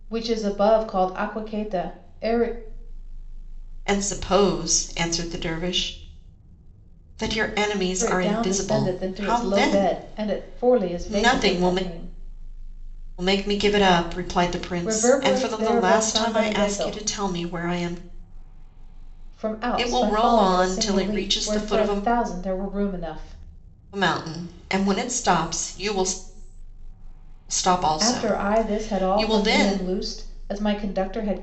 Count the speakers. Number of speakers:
2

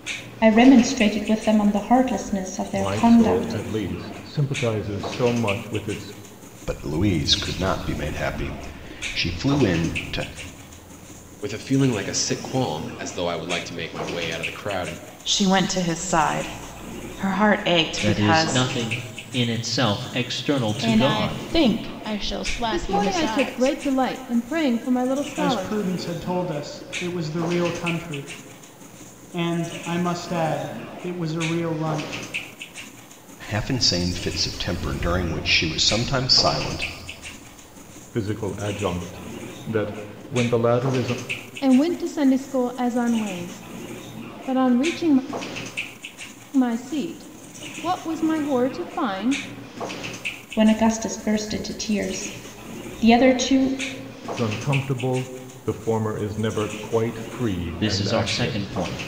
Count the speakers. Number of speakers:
9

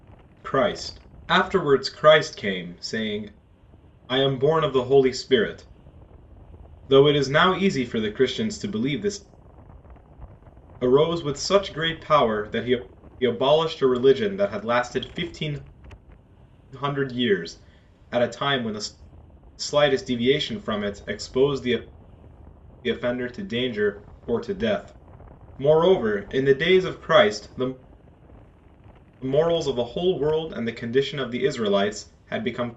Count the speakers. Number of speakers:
1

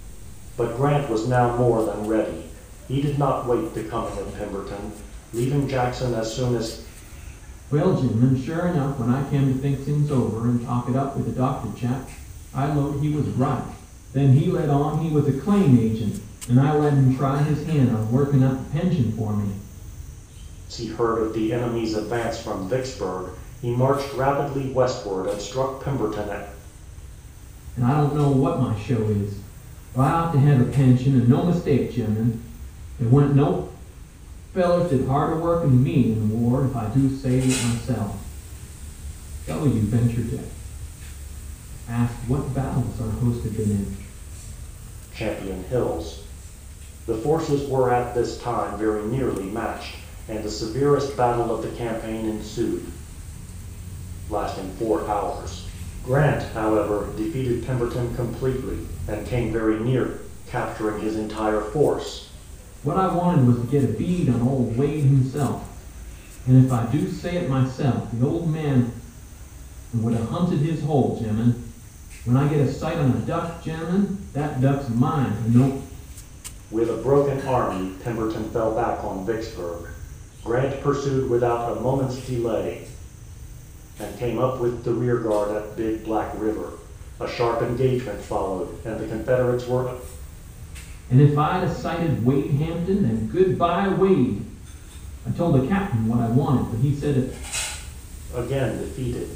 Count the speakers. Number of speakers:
2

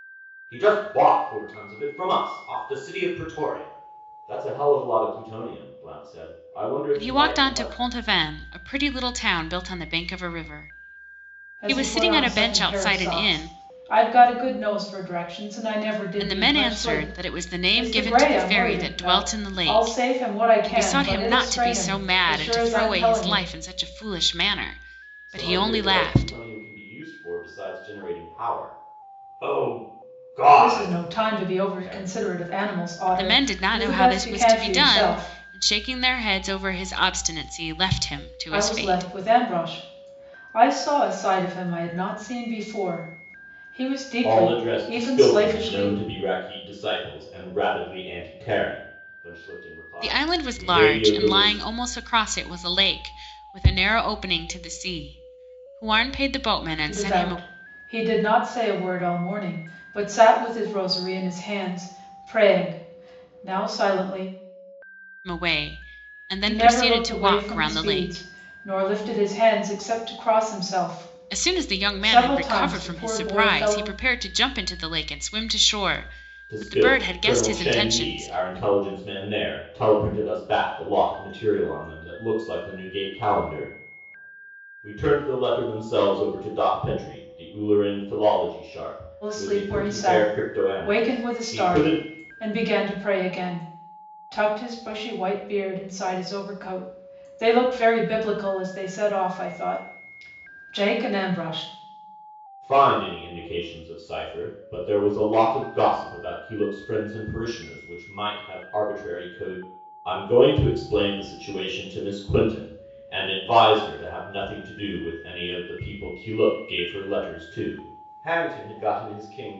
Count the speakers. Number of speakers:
3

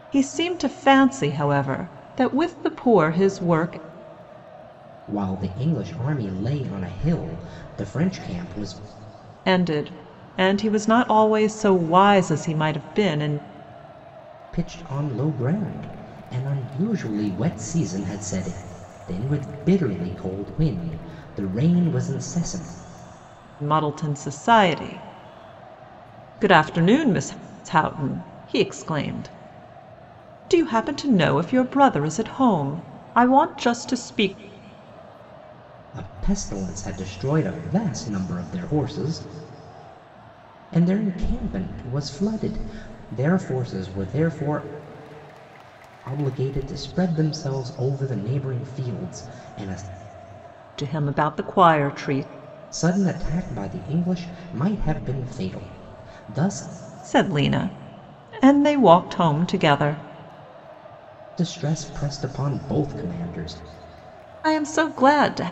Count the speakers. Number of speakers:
2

